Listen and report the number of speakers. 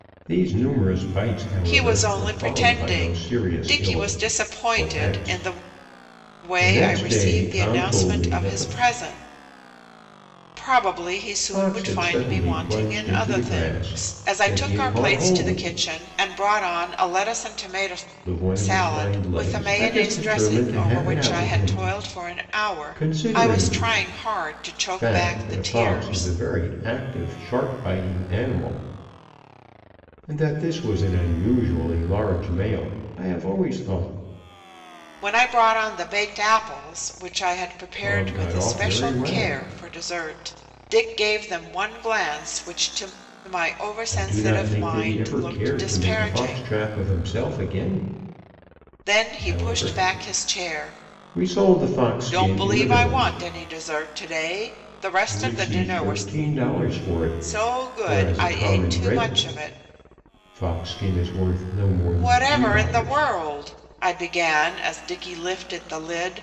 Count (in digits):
2